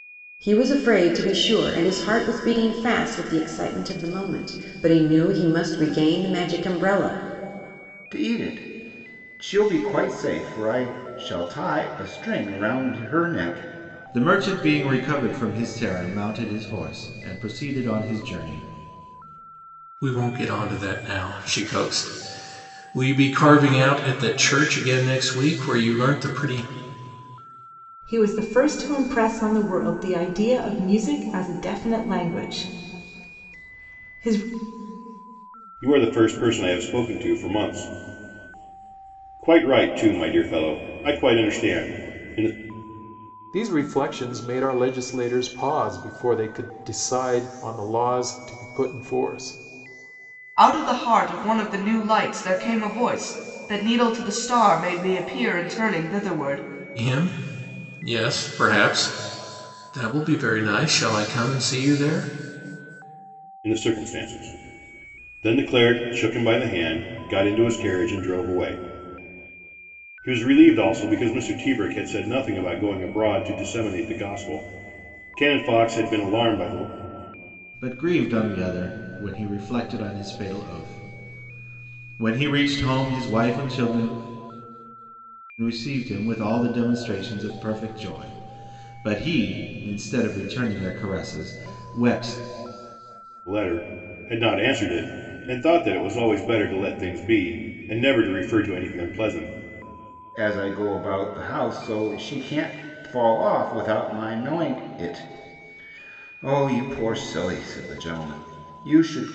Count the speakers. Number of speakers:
8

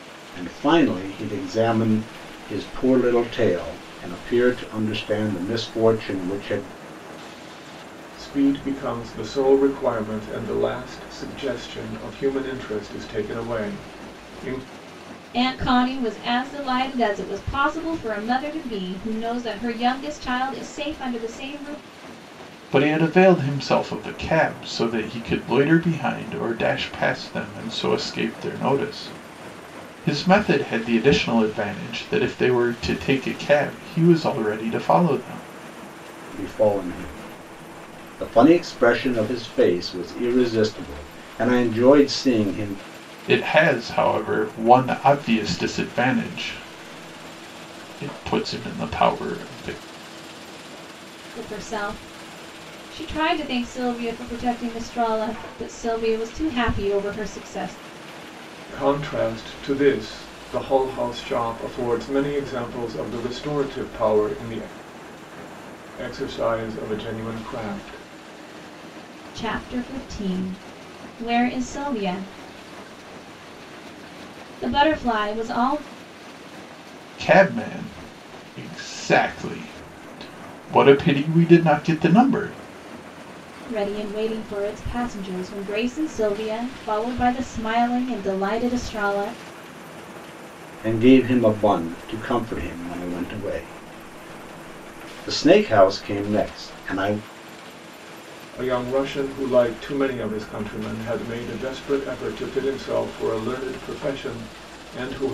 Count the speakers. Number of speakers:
4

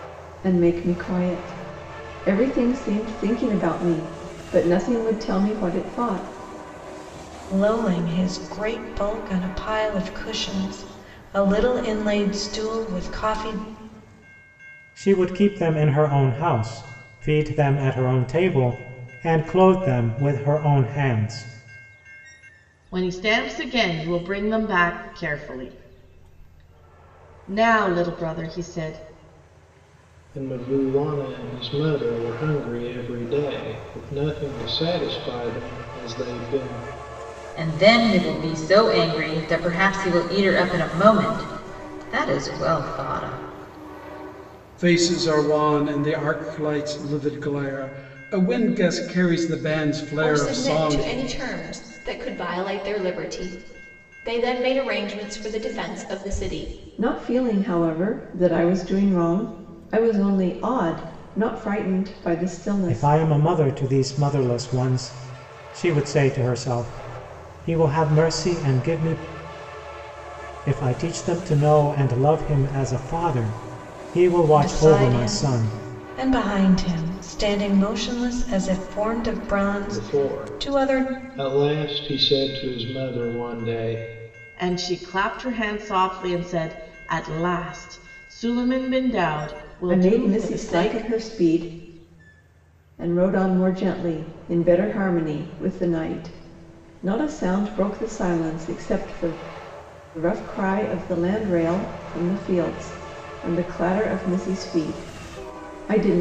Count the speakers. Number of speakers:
8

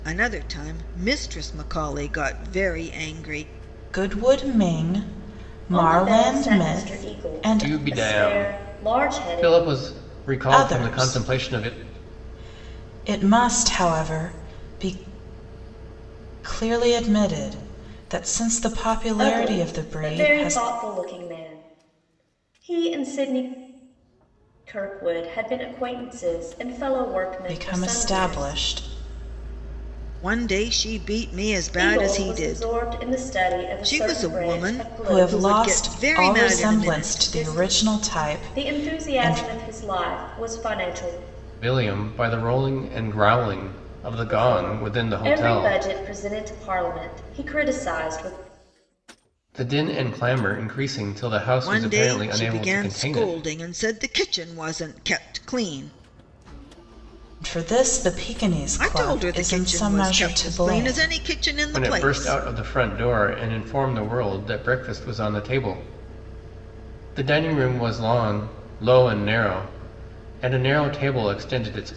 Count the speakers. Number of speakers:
4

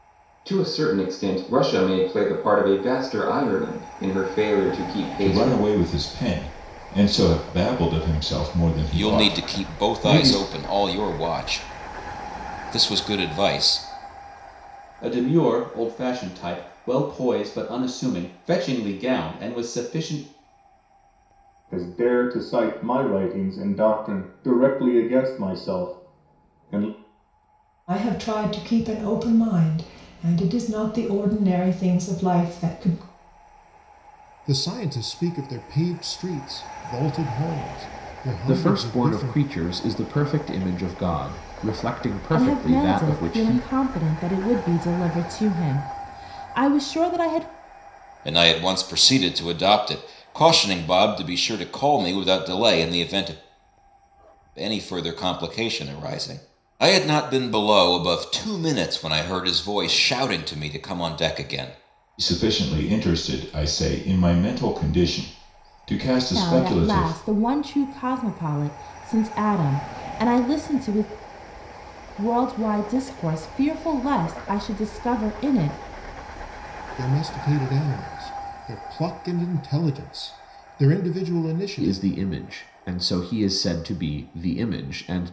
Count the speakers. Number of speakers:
9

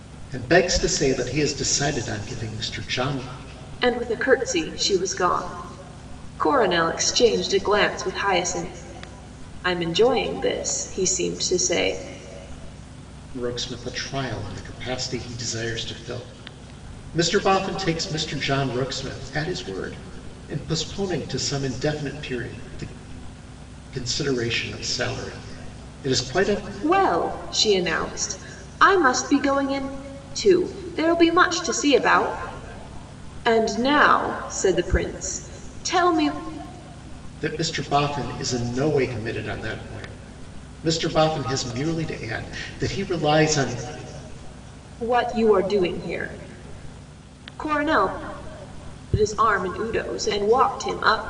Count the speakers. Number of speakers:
2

